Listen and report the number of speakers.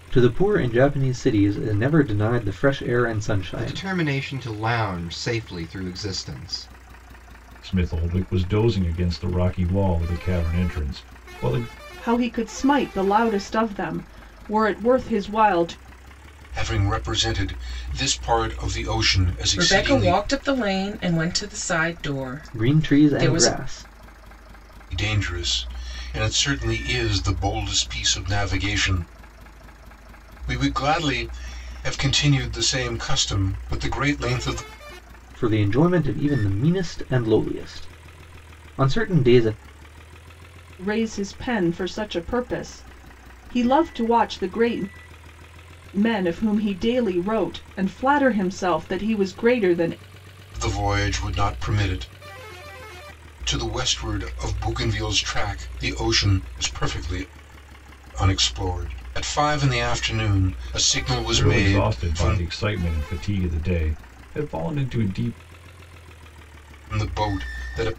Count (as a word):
six